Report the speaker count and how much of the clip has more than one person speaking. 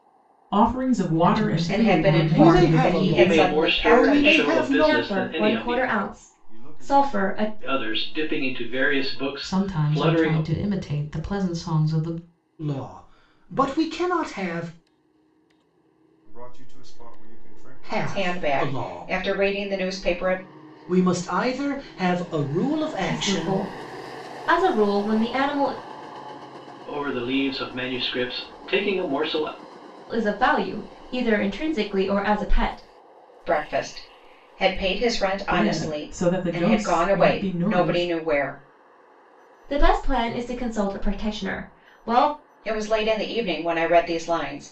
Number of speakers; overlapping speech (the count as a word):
seven, about 28%